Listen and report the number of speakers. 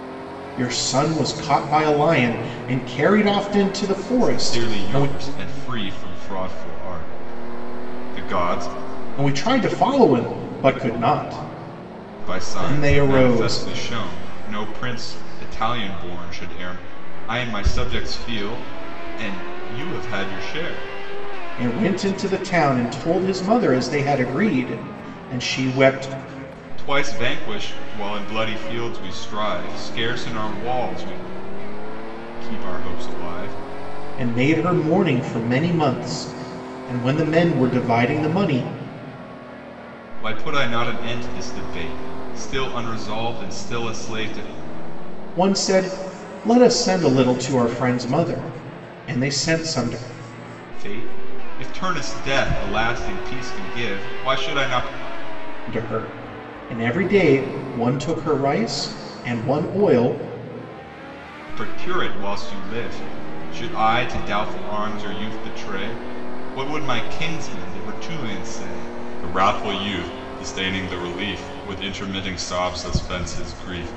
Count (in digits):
2